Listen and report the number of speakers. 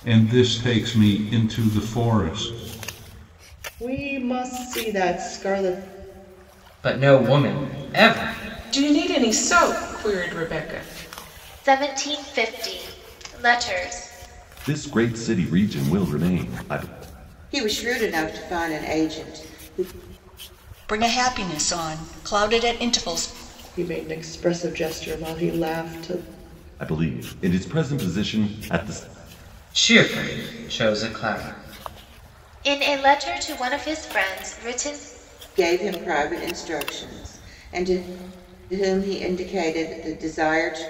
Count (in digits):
8